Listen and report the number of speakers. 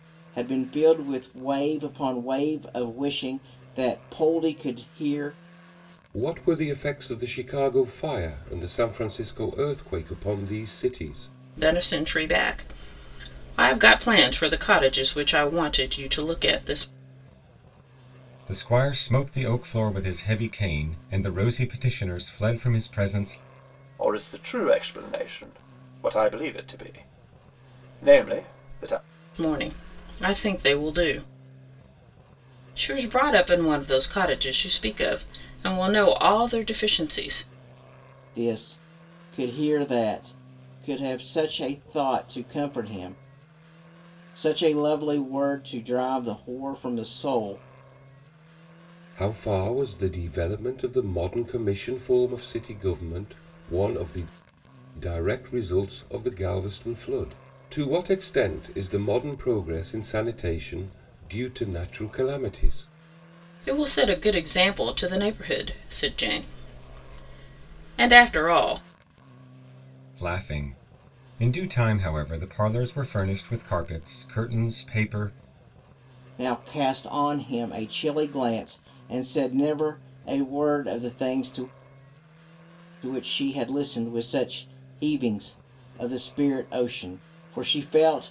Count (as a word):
five